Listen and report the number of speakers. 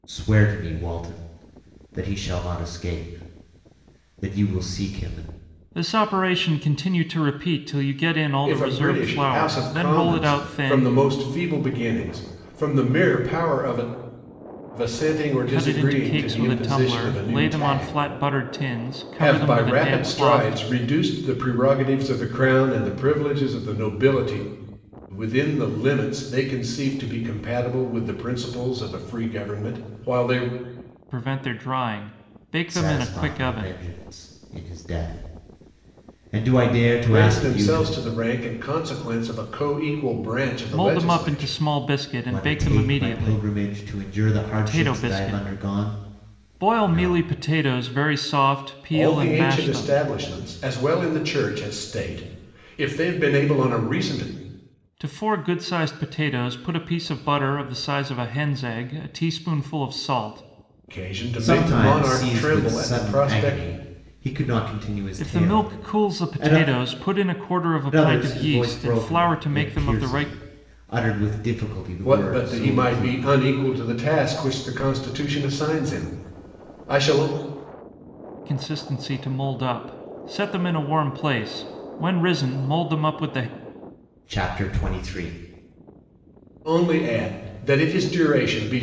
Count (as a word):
three